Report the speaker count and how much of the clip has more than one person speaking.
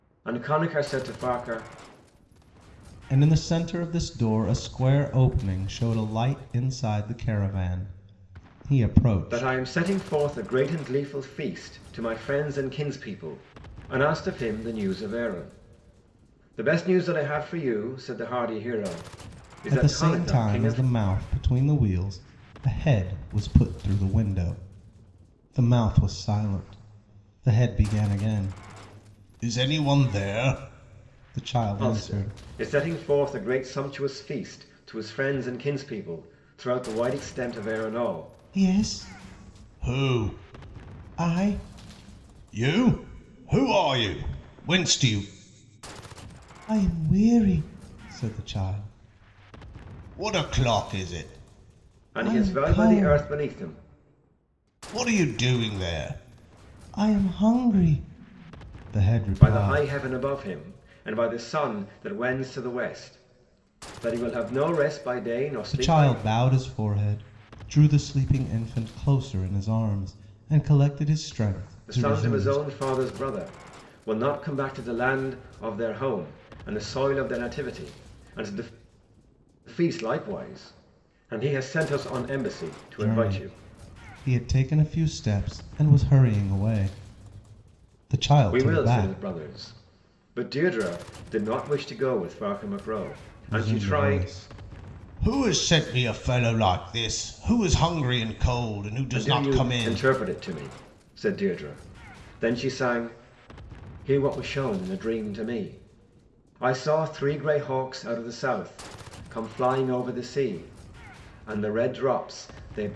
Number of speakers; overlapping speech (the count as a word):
two, about 8%